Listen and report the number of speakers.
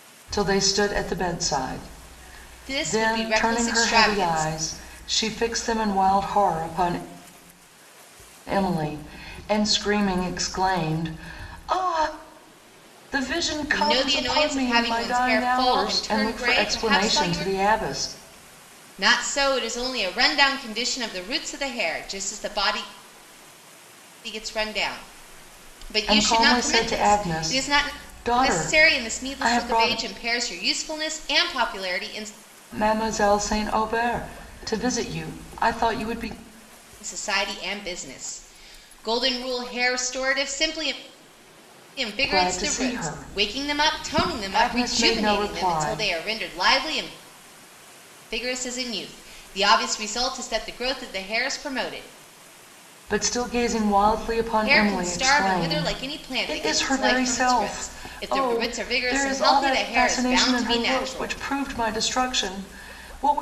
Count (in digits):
2